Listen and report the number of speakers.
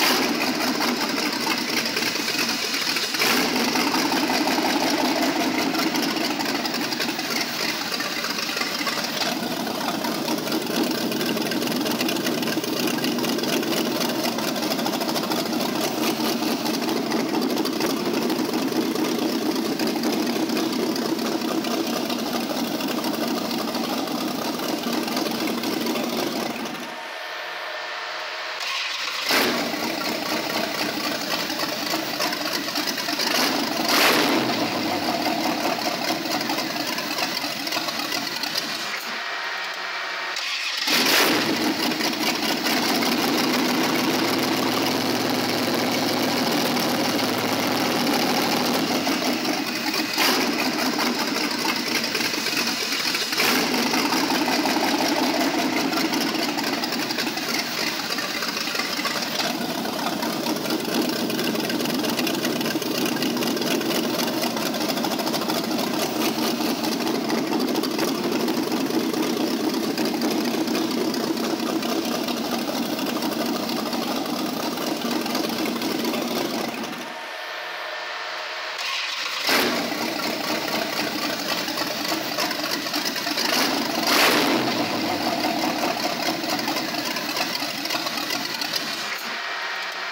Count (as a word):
zero